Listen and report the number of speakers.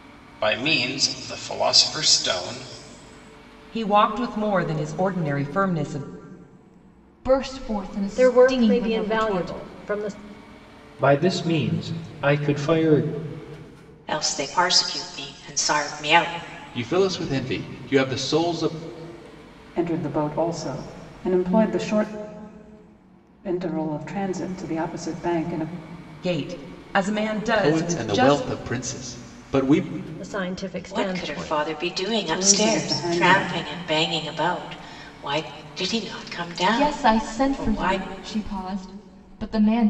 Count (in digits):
8